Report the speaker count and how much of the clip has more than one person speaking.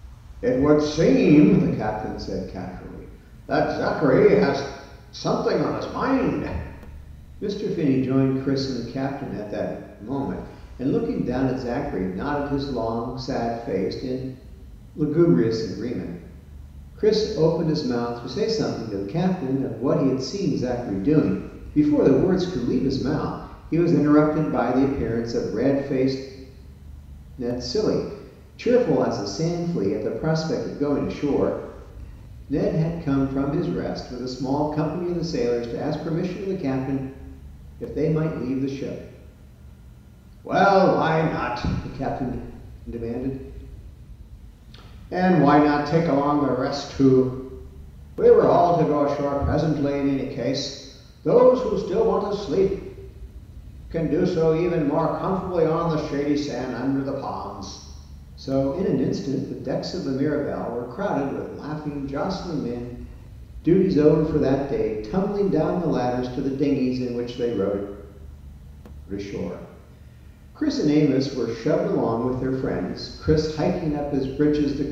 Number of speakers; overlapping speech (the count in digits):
1, no overlap